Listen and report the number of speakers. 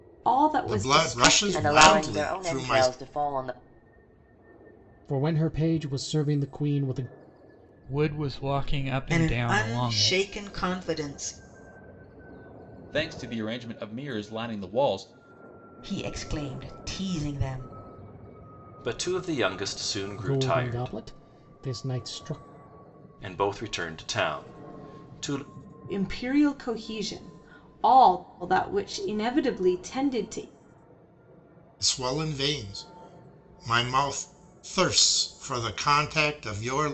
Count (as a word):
nine